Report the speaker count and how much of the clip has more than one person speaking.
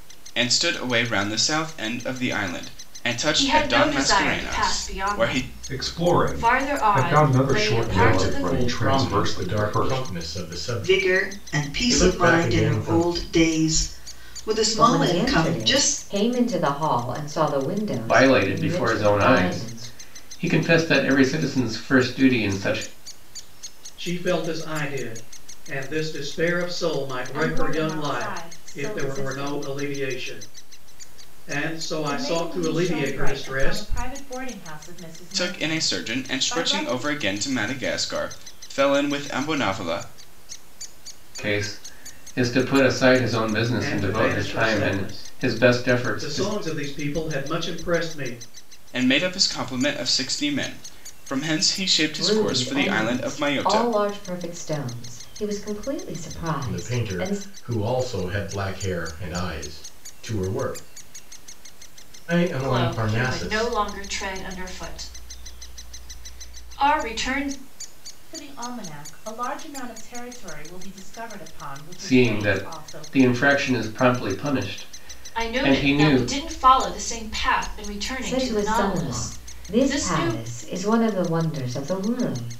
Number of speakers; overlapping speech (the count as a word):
nine, about 35%